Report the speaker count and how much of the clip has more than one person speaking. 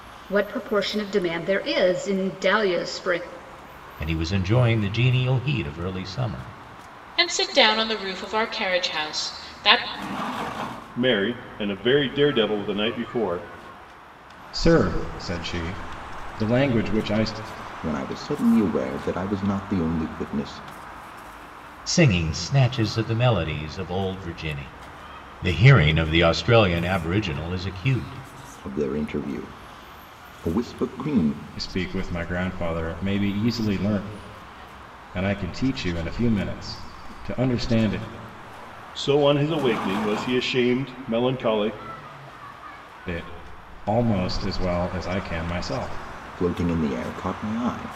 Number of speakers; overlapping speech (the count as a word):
six, no overlap